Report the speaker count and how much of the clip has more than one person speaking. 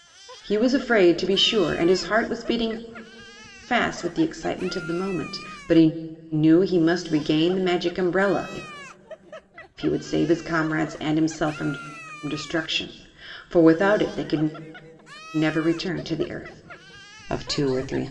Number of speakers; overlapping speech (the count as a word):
one, no overlap